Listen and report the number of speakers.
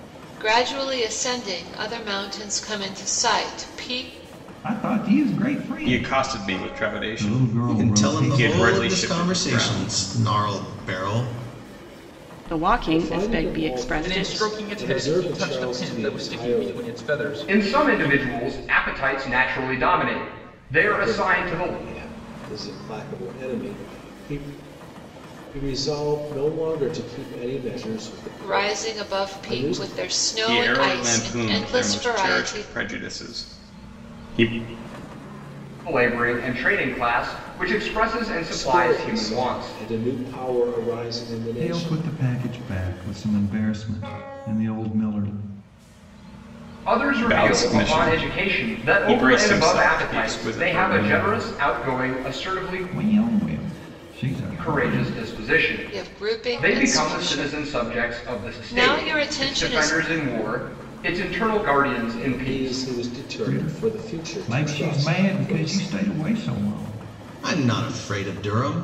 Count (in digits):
8